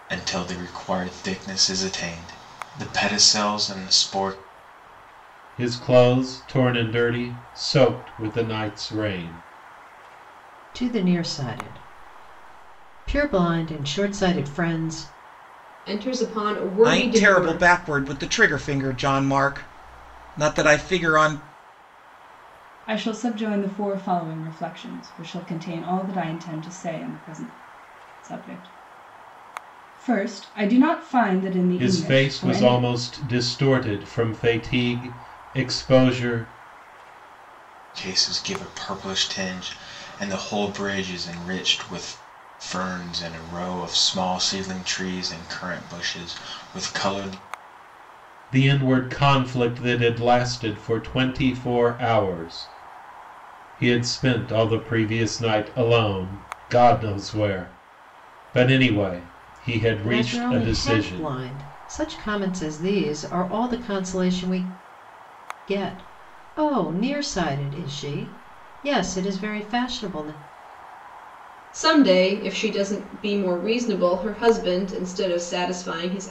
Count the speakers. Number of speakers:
six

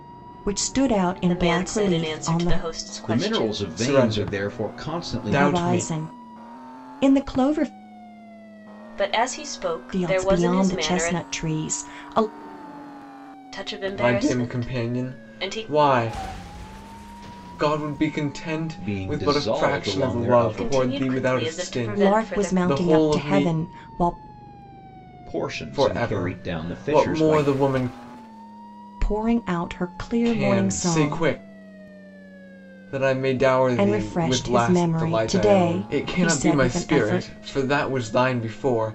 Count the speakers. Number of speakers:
four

